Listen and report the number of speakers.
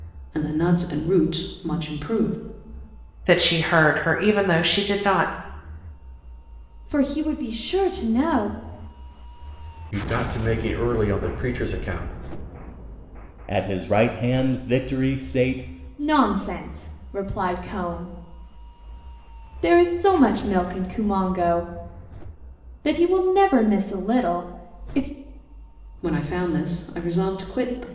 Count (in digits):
5